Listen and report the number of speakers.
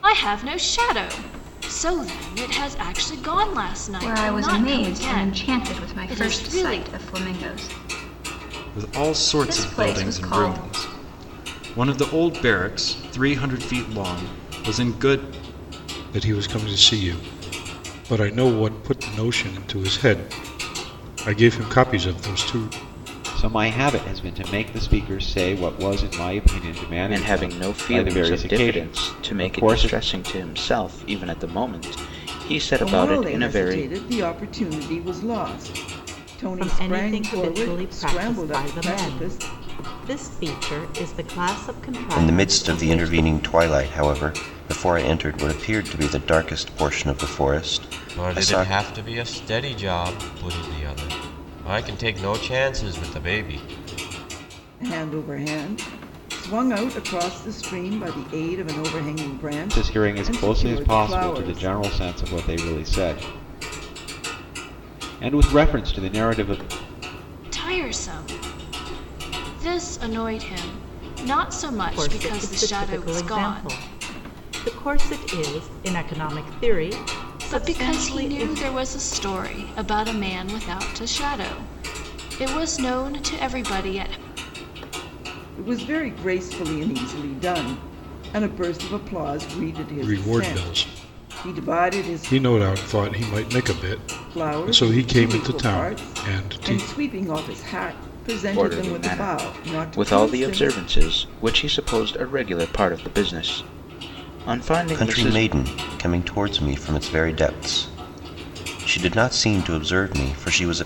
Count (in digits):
10